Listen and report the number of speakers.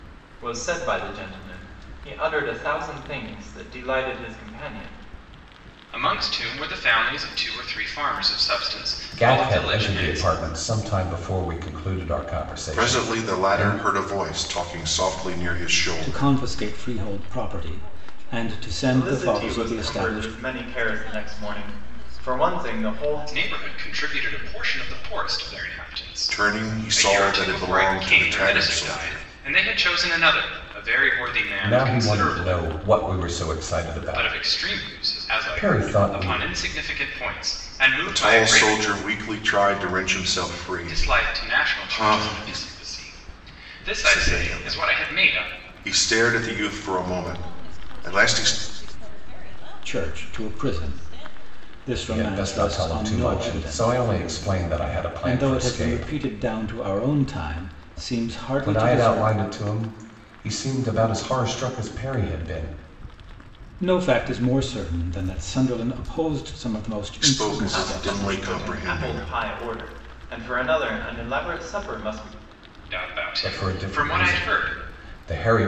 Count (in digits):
6